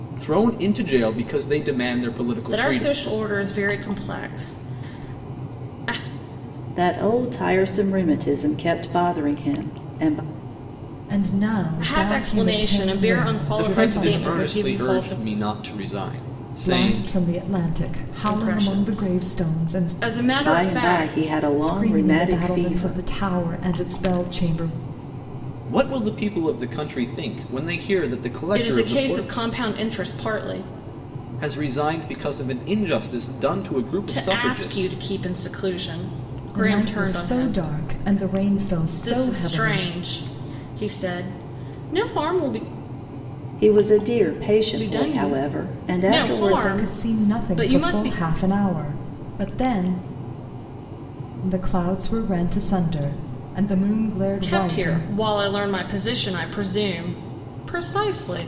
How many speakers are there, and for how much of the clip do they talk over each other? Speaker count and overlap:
4, about 28%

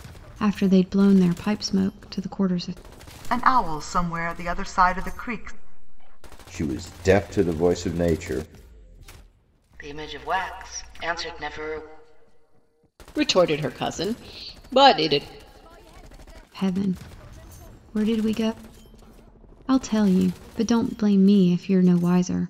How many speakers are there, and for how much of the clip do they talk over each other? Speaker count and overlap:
5, no overlap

